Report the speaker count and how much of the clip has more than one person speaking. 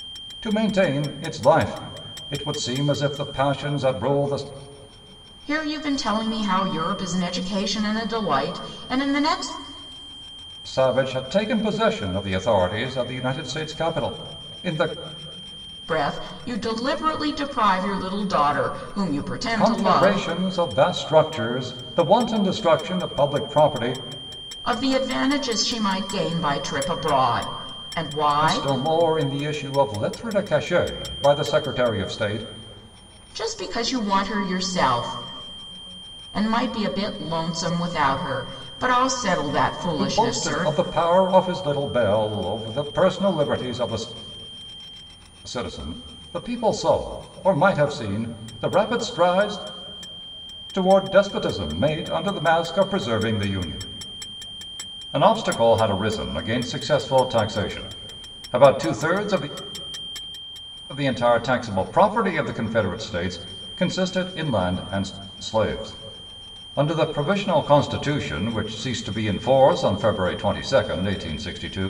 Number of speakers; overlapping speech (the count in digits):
2, about 3%